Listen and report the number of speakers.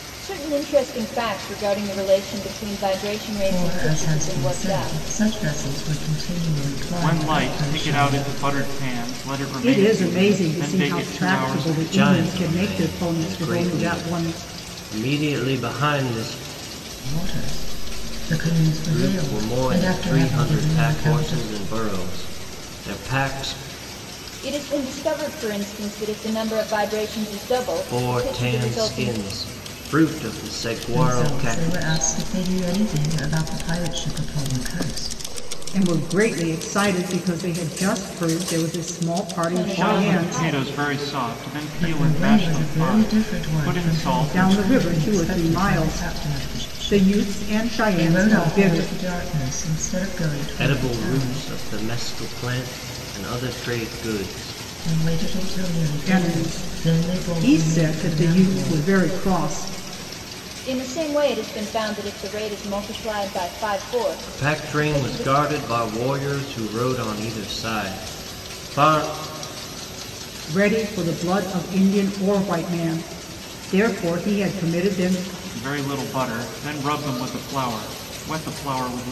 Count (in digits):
5